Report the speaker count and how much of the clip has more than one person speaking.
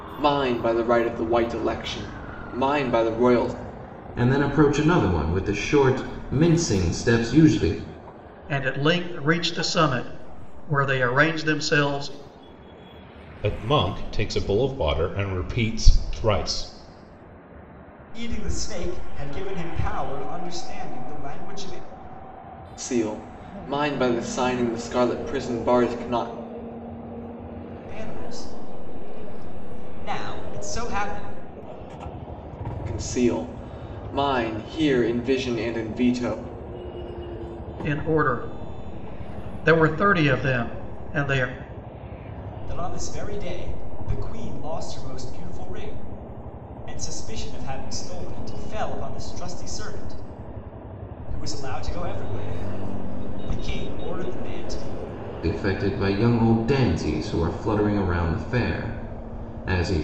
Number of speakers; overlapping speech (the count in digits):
5, no overlap